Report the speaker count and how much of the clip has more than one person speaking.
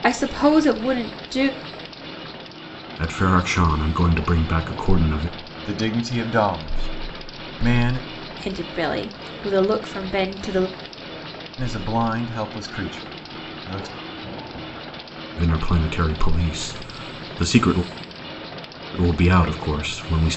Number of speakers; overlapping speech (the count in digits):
3, no overlap